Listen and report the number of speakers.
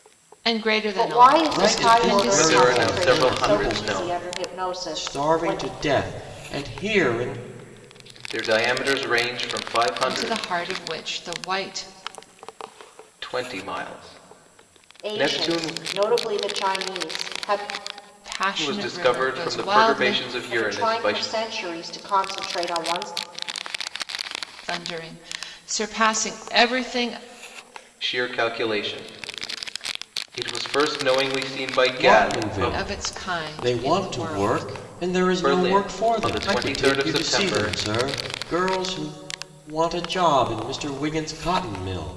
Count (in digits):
4